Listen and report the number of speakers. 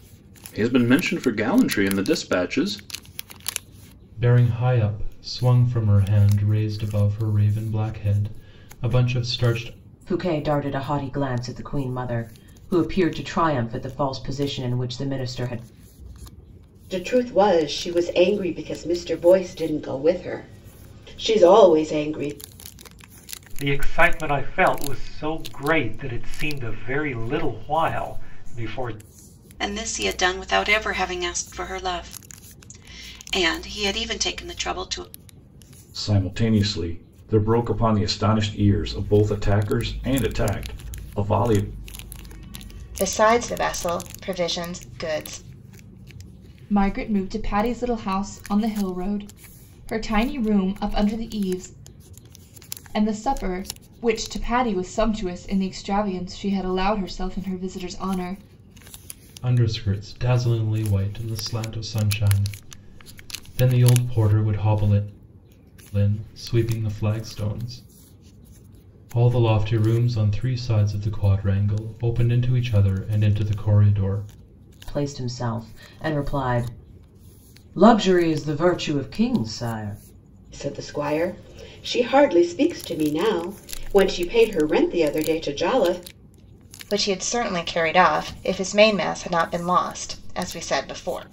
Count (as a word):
nine